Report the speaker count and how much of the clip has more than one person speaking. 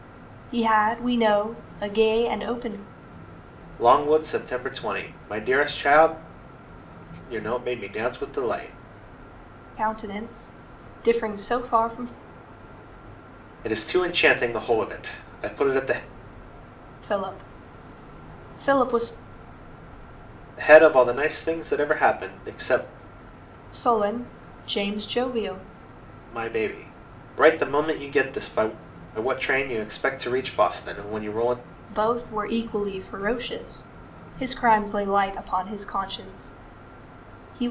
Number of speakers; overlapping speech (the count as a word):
two, no overlap